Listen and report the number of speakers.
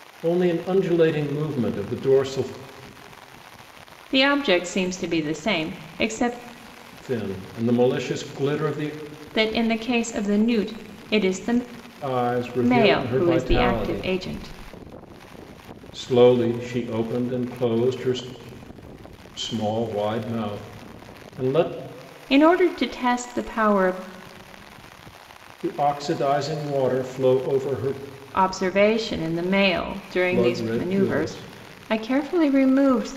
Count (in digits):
2